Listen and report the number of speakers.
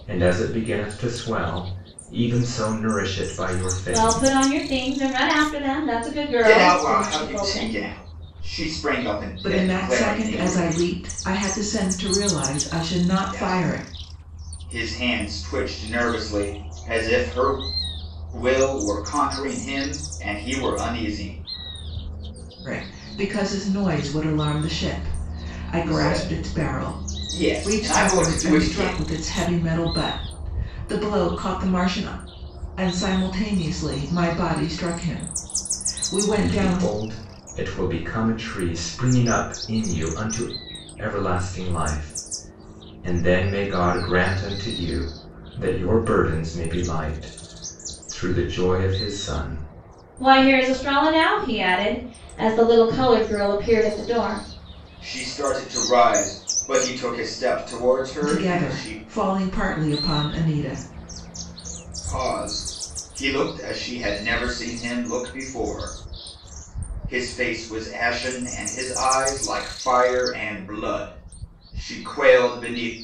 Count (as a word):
four